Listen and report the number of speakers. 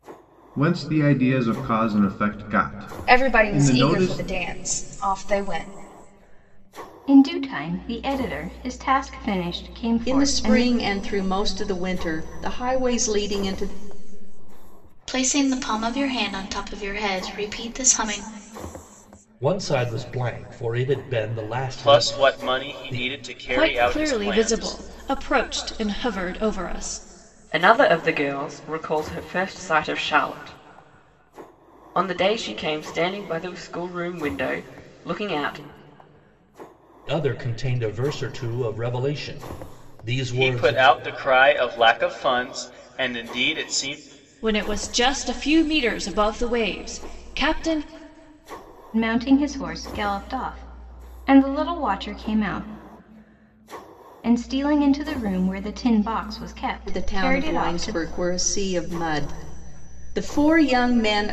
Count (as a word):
nine